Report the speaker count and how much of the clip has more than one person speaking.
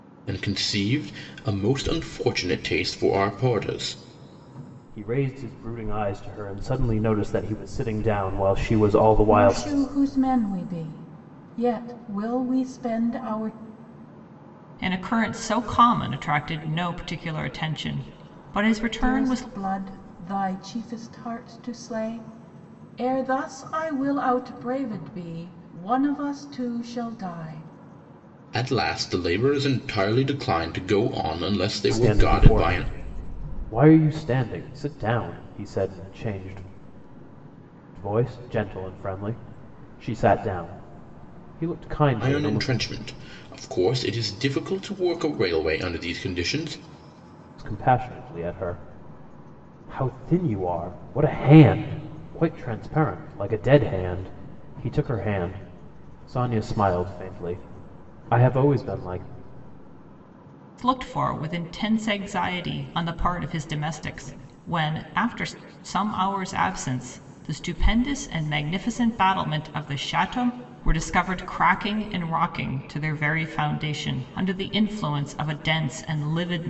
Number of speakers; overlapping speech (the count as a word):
four, about 3%